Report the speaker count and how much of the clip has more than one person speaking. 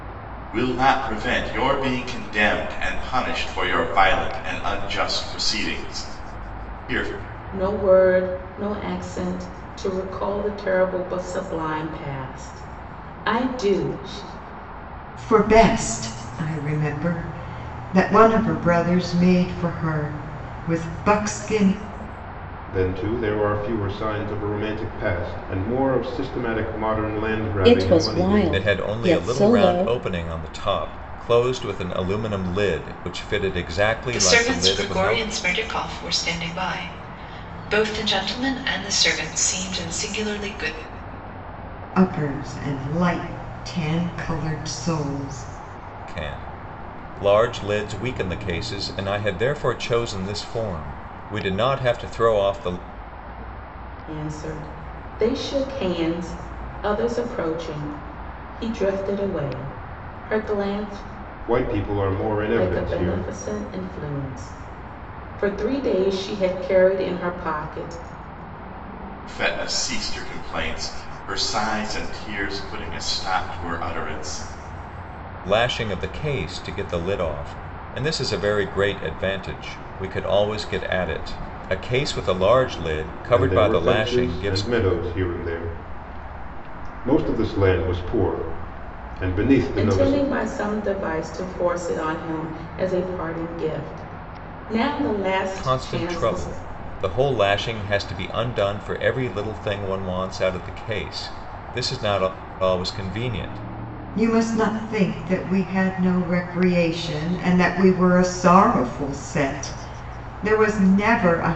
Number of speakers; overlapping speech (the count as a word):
seven, about 7%